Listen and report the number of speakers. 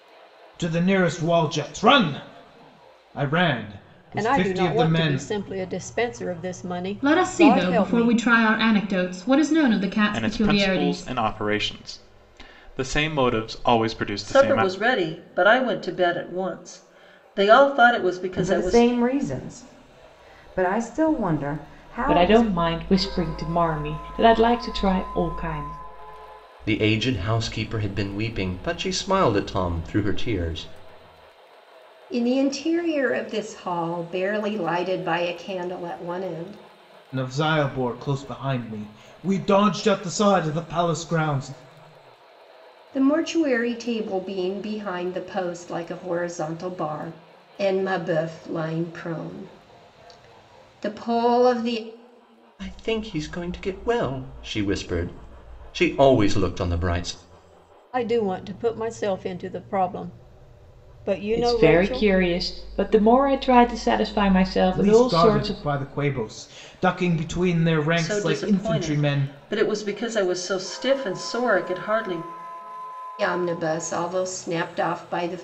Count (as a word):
nine